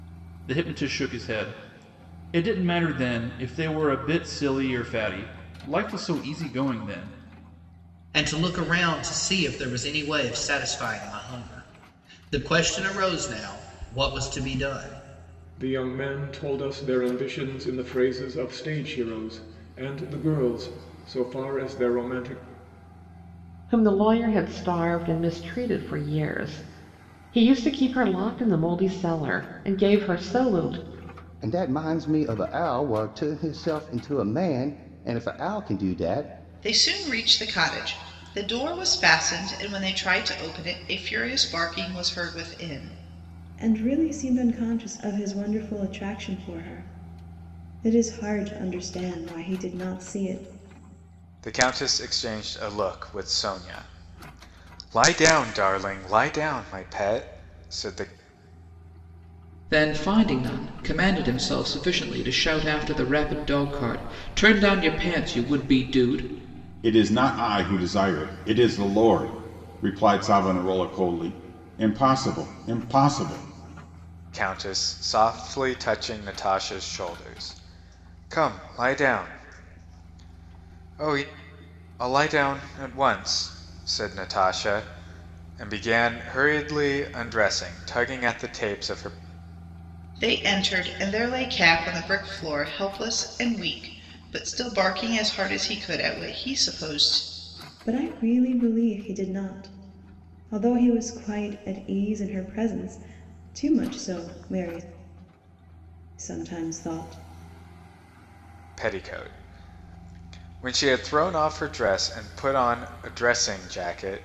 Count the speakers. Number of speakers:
10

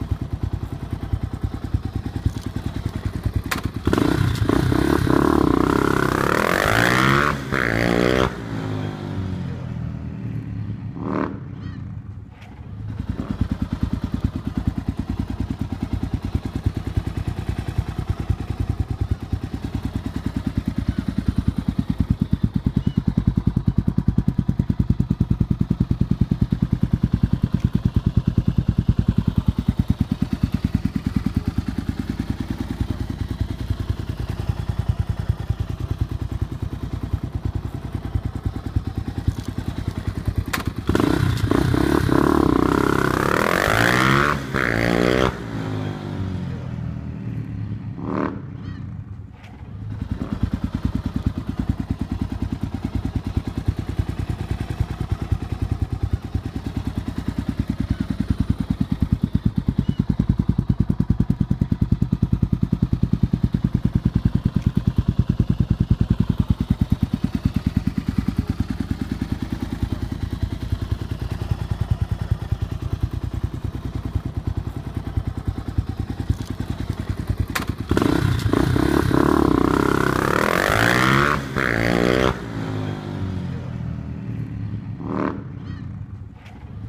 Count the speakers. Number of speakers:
0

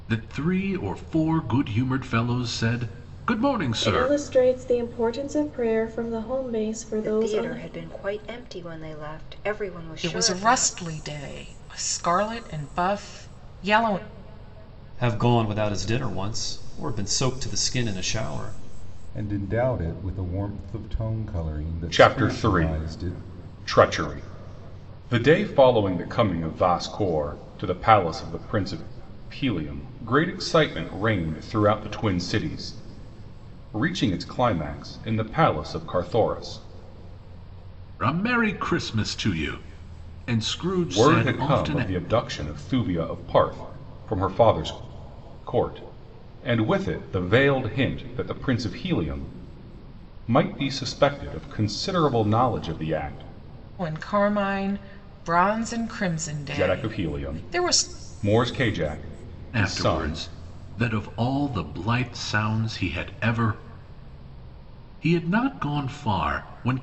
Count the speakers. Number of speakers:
7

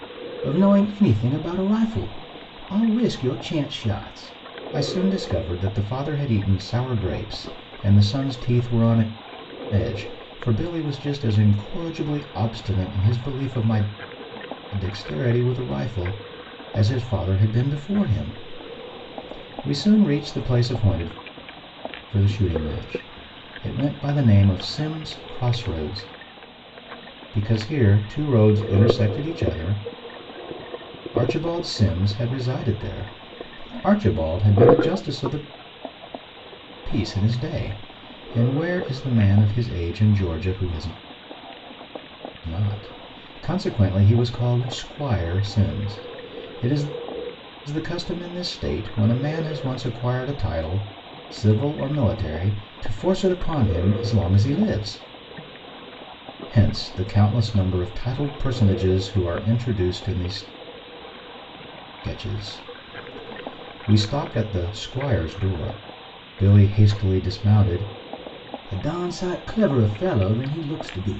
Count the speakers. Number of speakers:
1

